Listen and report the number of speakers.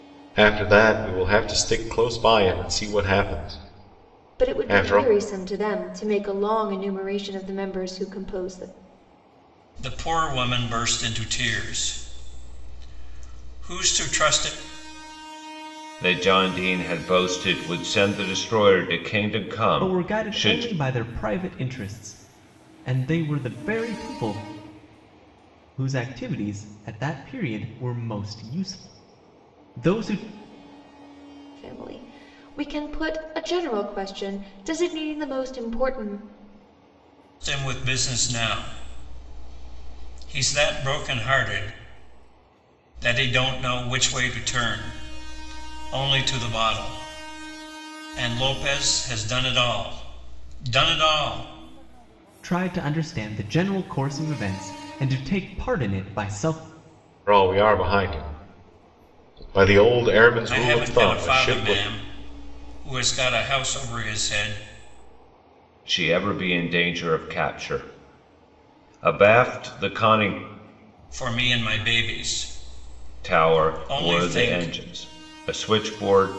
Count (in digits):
5